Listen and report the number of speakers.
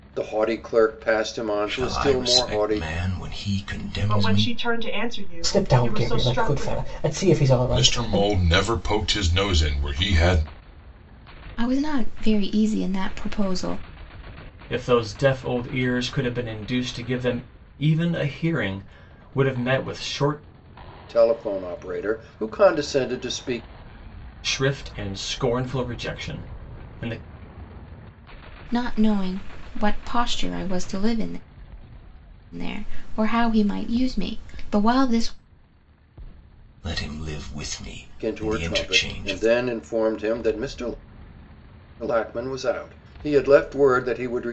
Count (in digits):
7